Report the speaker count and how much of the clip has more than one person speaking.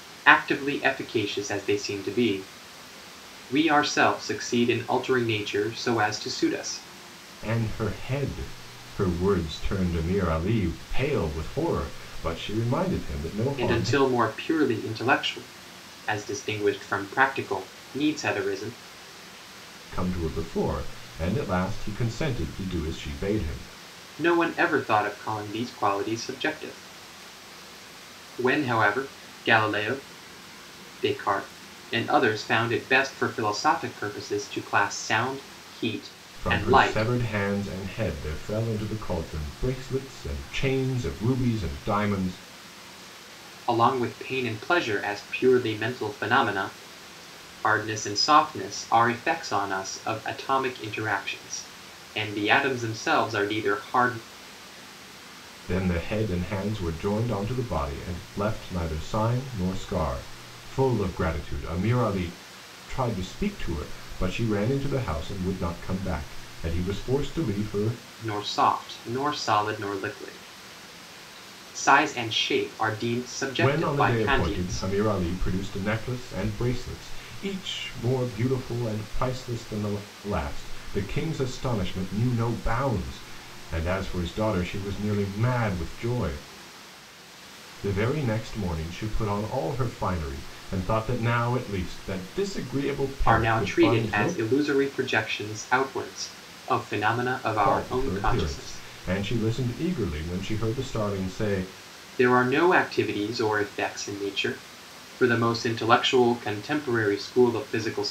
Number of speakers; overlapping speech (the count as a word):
two, about 5%